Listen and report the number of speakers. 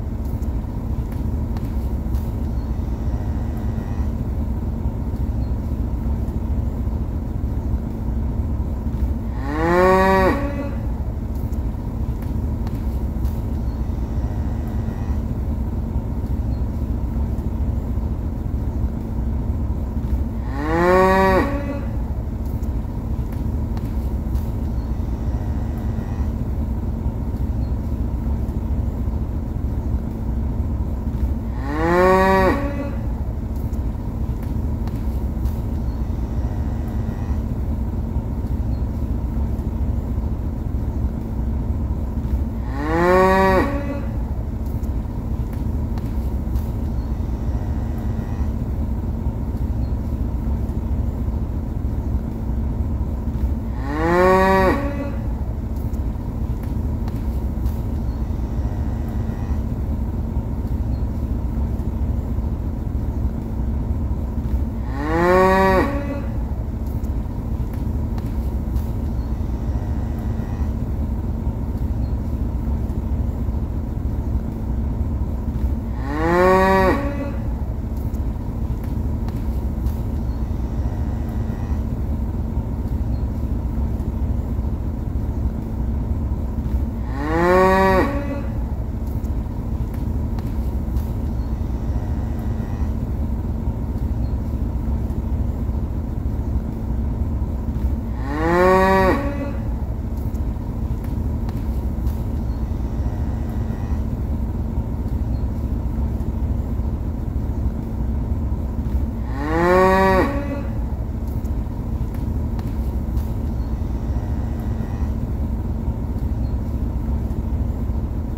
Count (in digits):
0